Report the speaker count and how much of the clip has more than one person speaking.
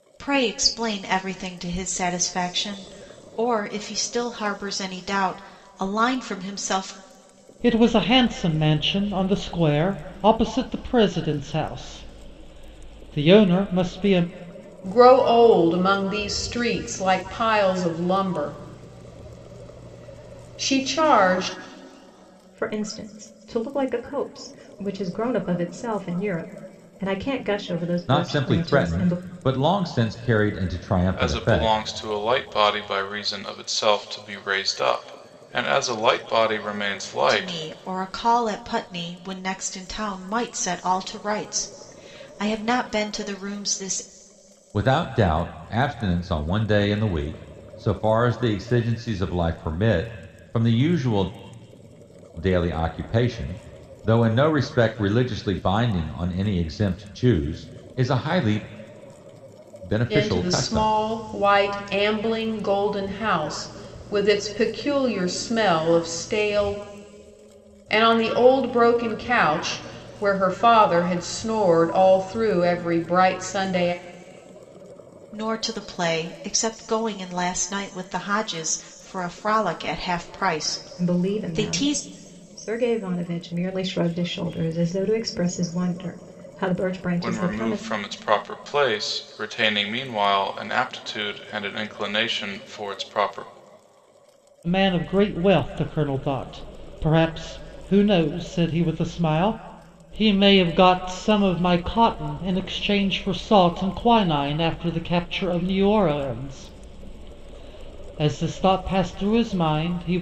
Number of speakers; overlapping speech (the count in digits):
6, about 4%